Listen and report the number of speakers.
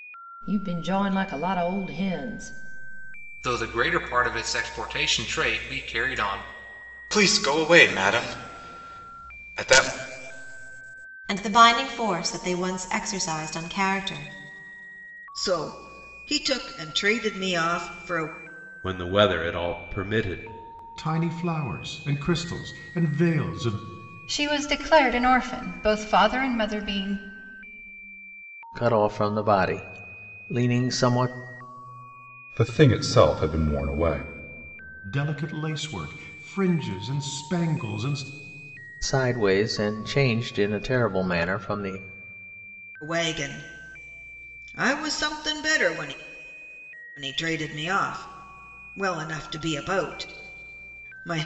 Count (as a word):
ten